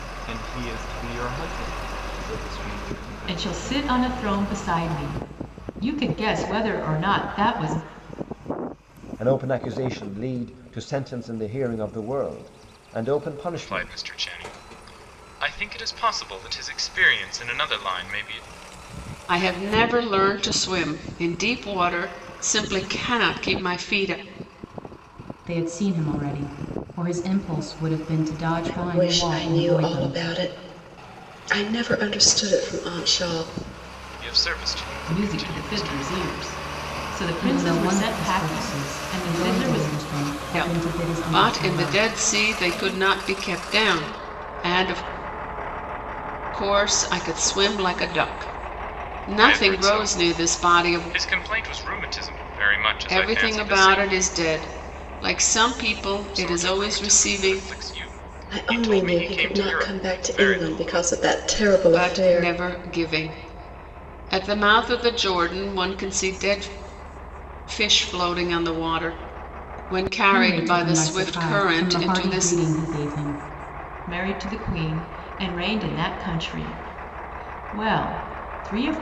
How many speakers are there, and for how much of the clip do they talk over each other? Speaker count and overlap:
seven, about 23%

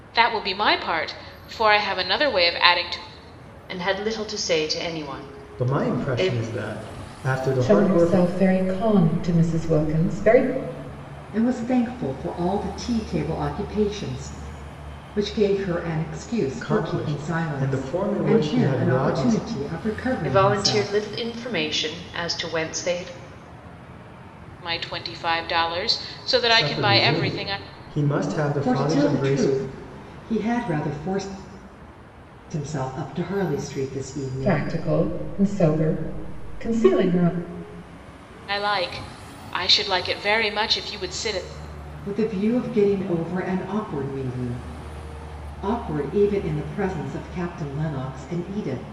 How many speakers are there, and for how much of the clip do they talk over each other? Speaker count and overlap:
five, about 15%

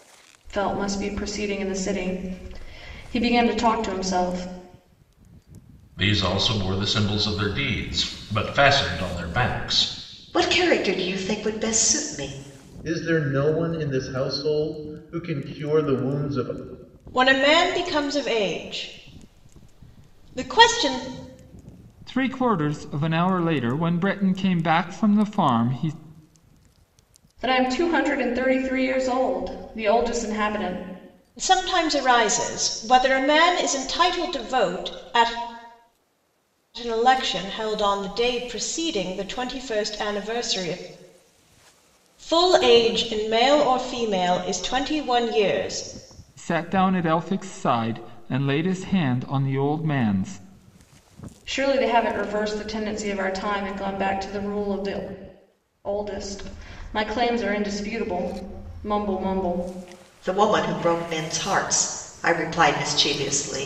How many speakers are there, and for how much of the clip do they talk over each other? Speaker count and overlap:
six, no overlap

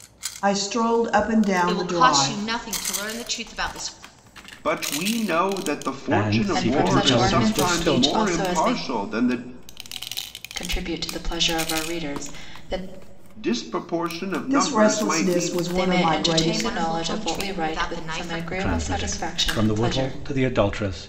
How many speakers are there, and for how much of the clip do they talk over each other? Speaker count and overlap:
five, about 44%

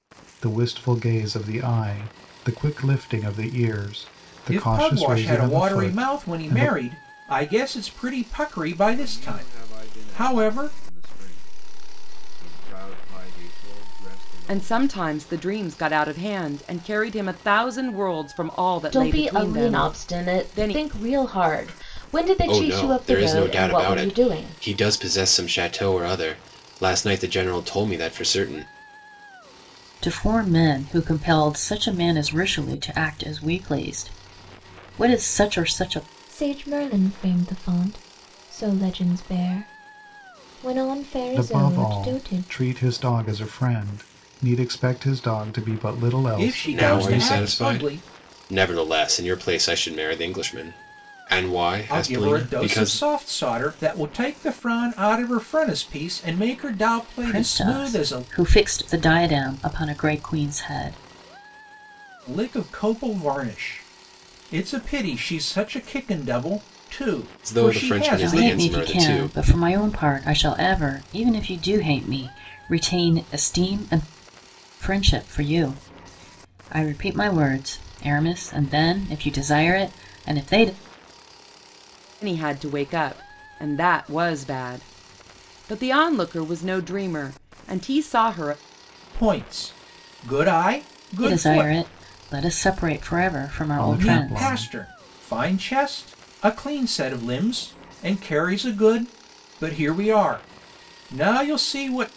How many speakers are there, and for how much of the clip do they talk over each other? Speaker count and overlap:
eight, about 17%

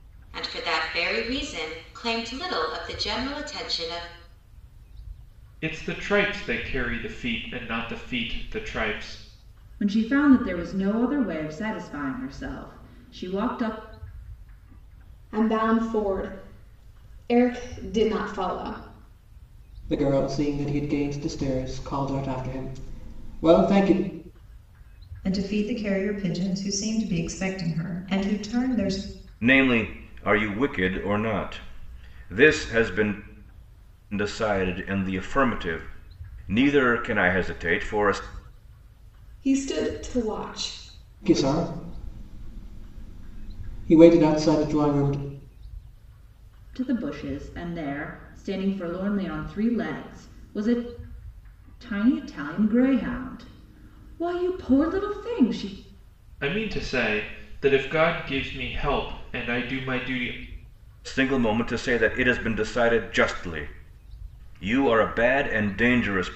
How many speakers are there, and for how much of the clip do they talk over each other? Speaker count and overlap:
seven, no overlap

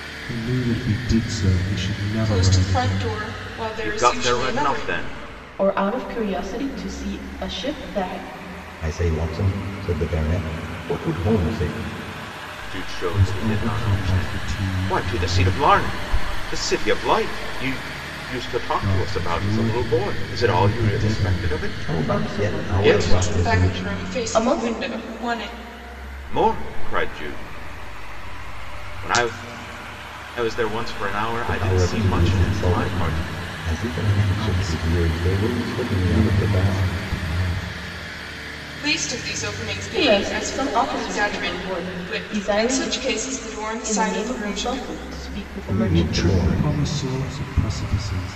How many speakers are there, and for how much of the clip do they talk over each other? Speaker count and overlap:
five, about 42%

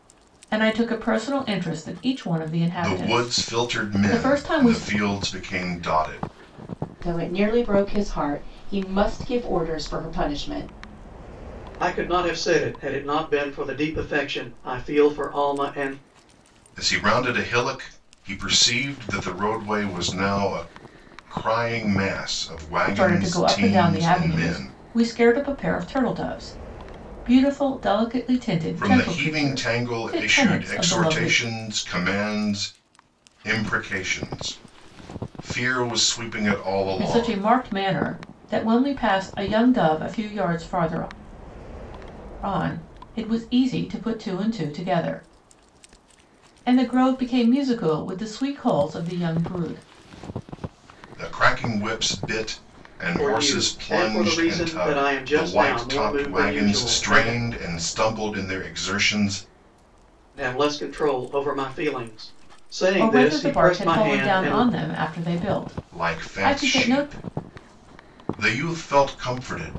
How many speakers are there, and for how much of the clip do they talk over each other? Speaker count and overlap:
four, about 20%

